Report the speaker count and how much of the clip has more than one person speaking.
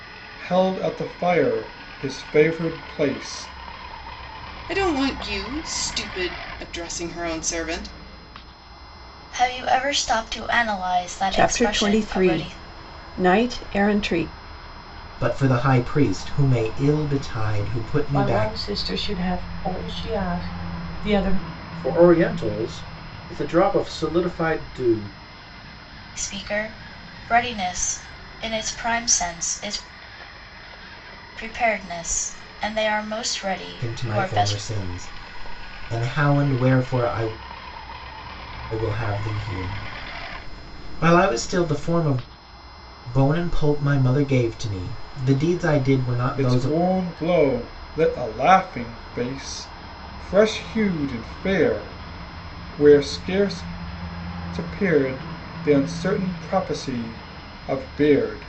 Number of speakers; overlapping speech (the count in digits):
7, about 5%